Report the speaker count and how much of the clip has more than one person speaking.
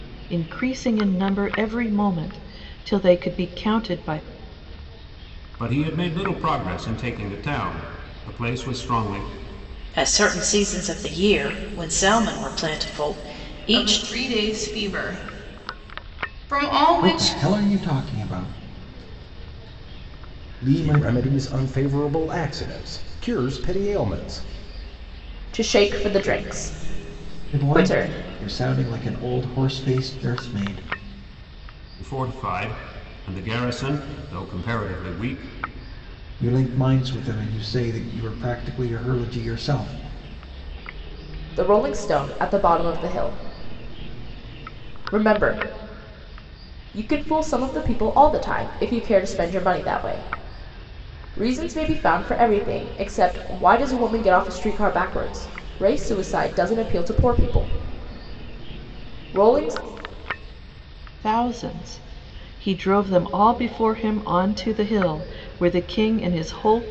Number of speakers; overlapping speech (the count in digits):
7, about 2%